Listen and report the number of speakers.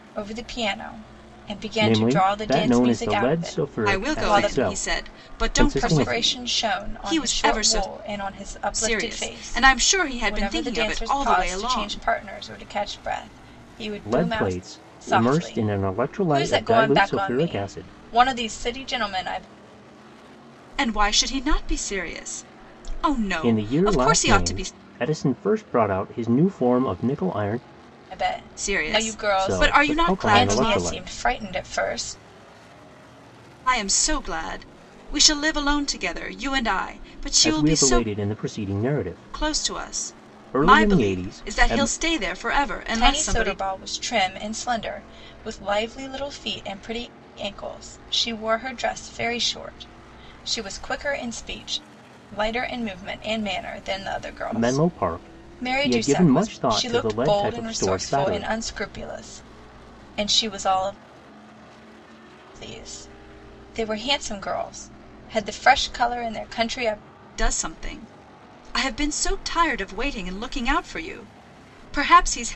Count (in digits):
3